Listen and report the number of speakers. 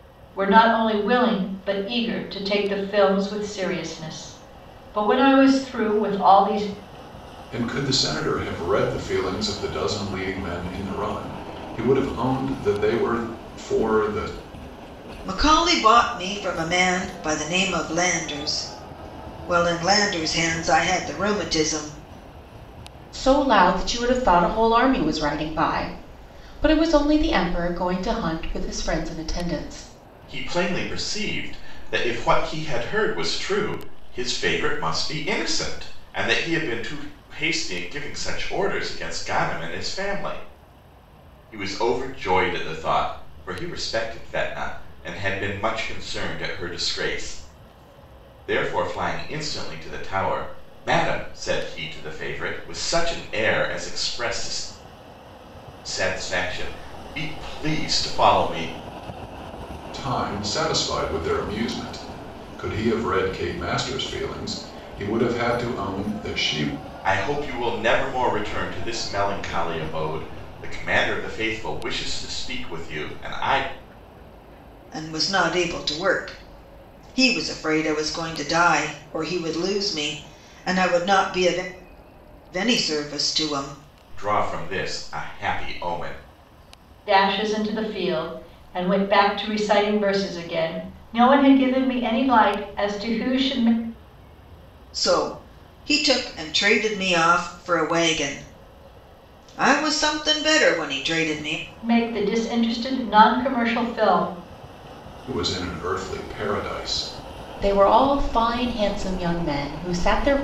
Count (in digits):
5